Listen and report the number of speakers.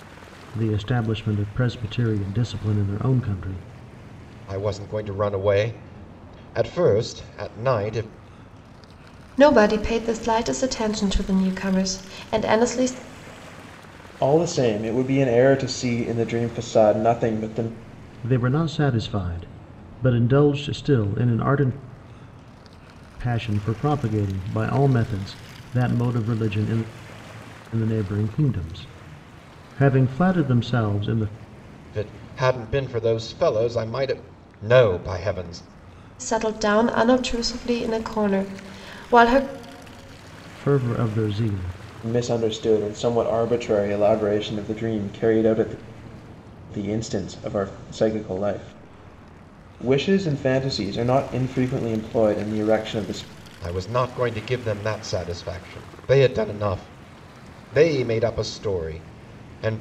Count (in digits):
4